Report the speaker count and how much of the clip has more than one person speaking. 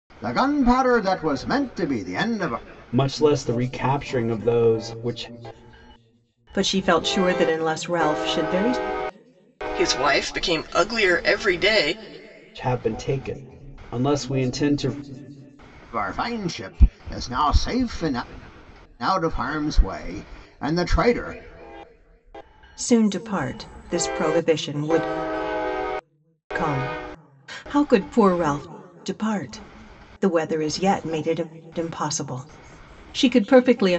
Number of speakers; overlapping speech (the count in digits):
4, no overlap